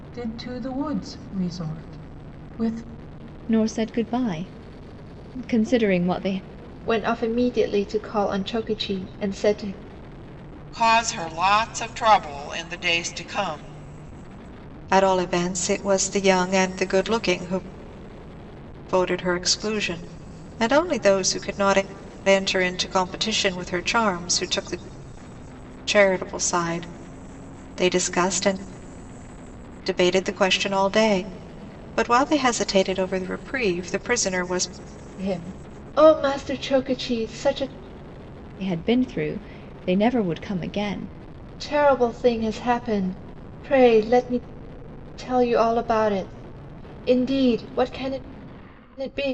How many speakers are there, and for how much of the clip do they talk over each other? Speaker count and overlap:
five, no overlap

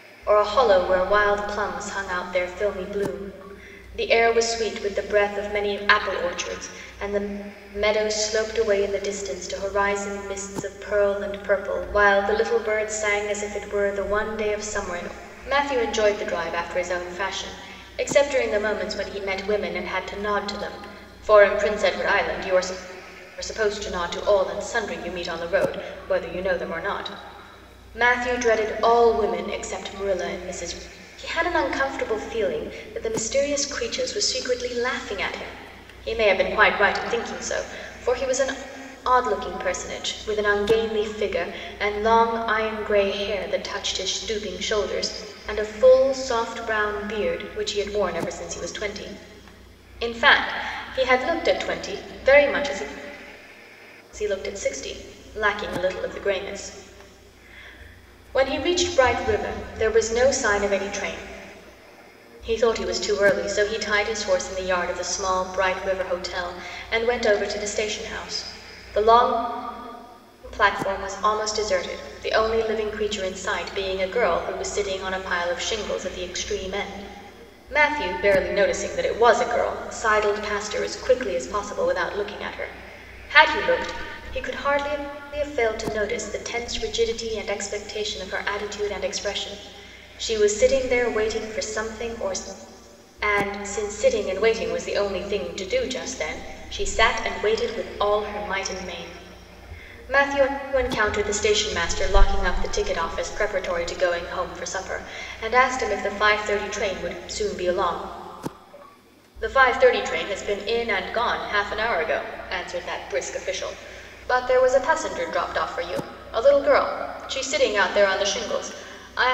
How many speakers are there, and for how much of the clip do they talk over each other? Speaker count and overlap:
one, no overlap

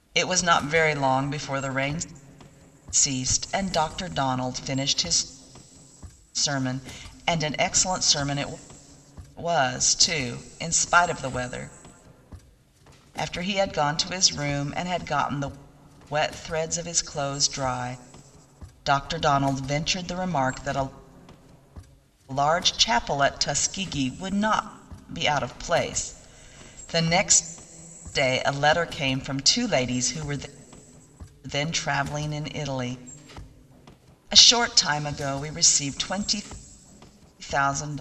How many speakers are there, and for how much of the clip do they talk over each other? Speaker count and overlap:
one, no overlap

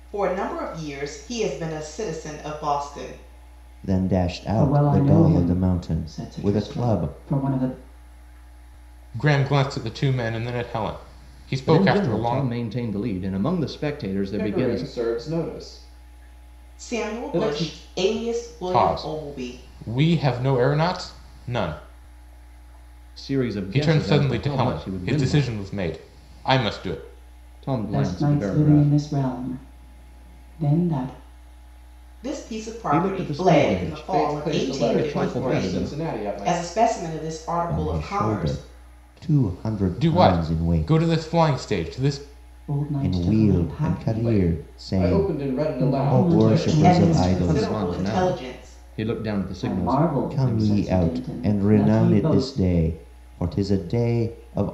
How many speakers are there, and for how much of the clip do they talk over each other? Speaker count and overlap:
six, about 45%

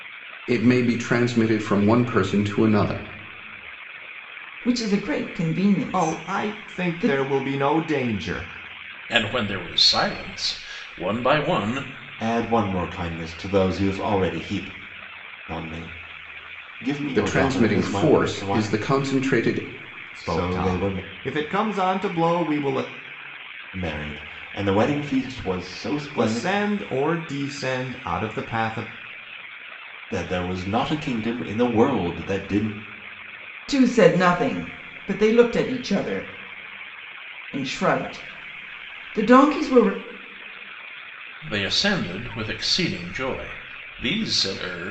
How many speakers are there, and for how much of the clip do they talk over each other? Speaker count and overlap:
five, about 11%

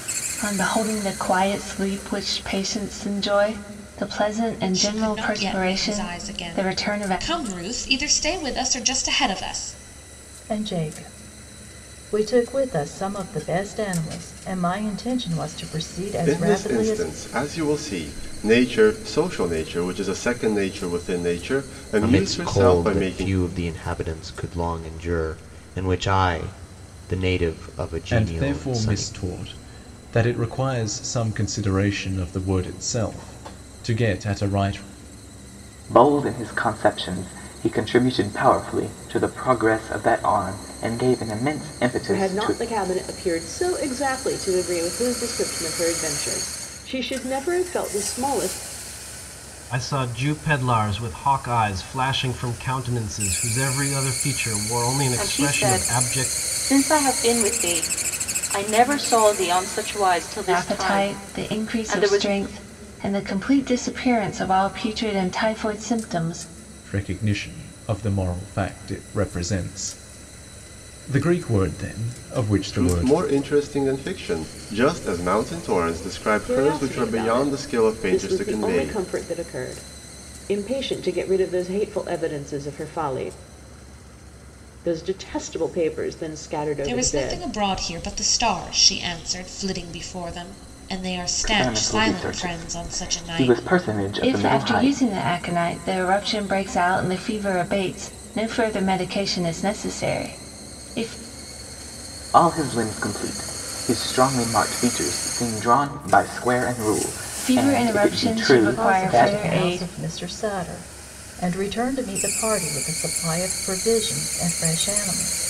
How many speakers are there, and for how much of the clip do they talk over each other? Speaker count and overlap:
ten, about 17%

